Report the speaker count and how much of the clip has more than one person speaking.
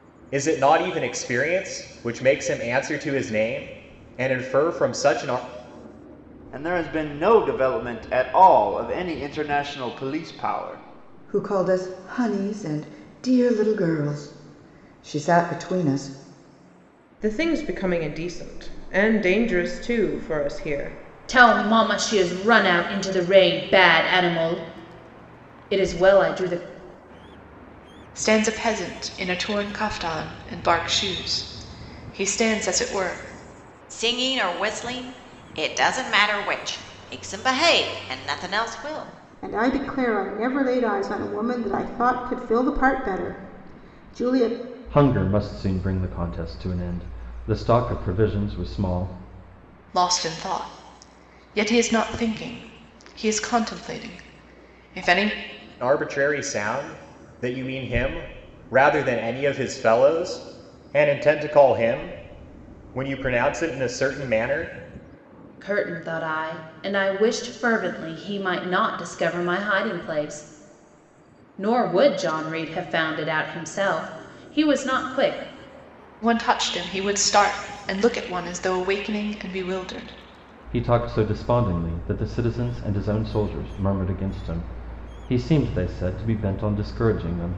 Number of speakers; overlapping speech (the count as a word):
nine, no overlap